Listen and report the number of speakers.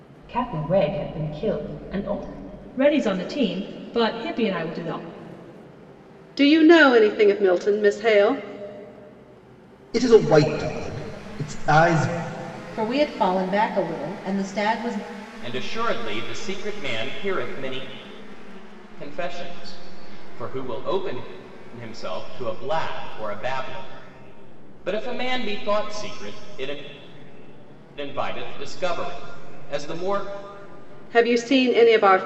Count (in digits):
6